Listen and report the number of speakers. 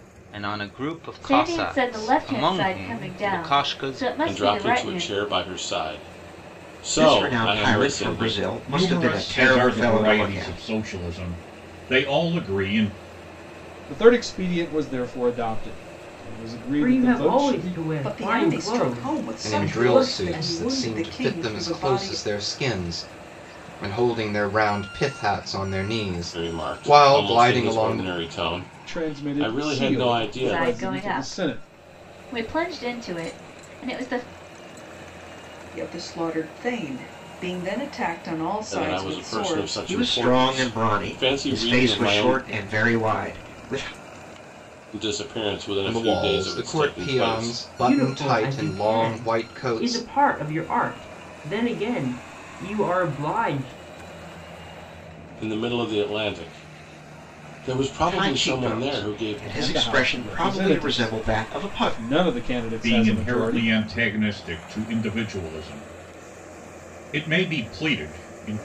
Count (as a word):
nine